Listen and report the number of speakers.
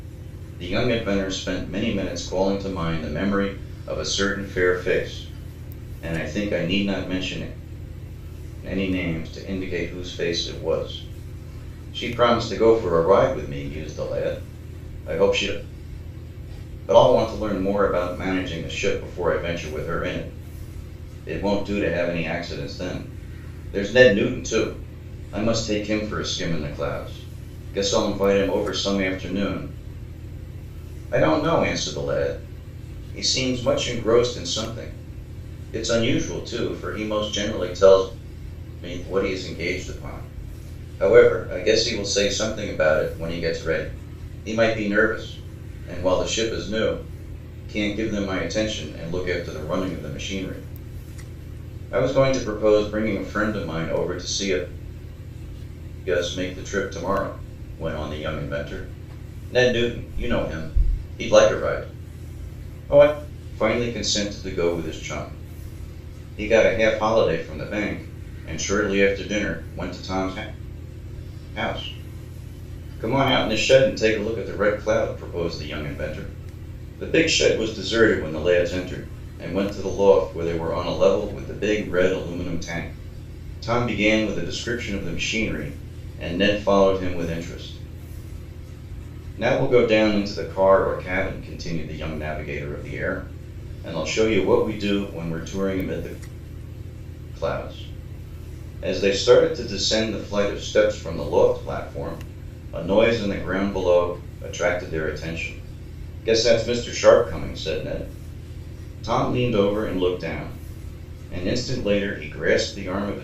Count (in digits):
1